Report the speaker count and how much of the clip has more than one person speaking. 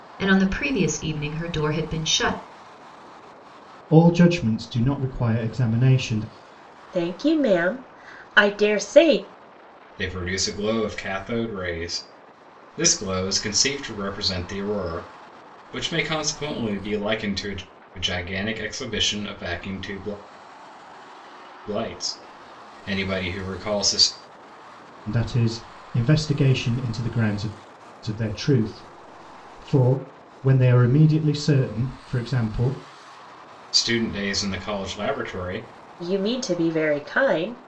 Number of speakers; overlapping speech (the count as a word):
four, no overlap